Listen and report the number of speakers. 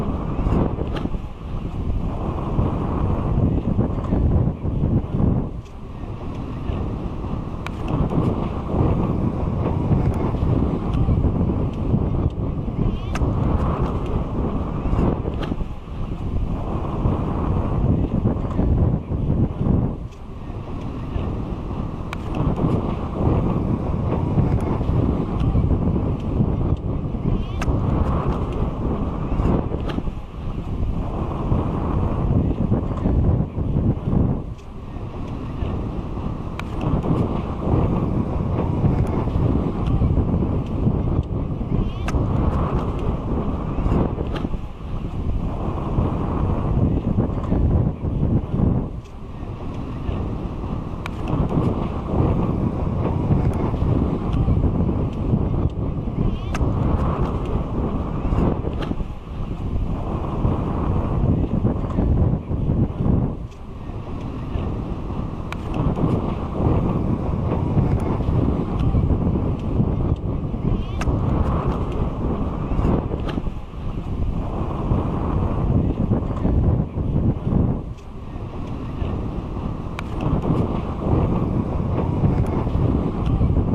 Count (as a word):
zero